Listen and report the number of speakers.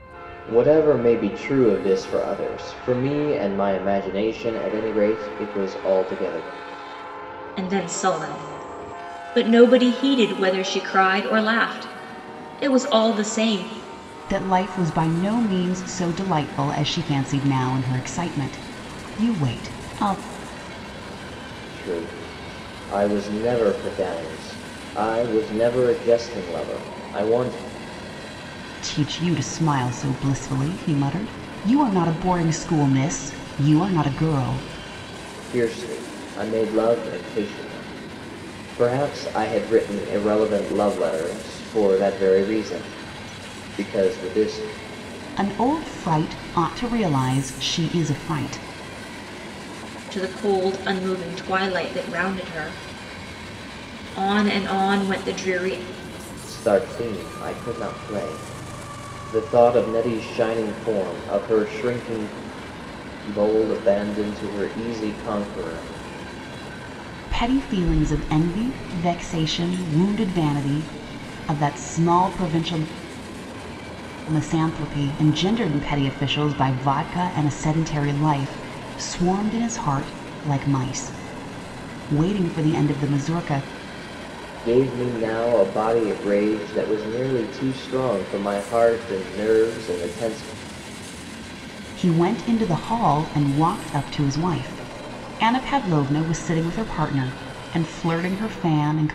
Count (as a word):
three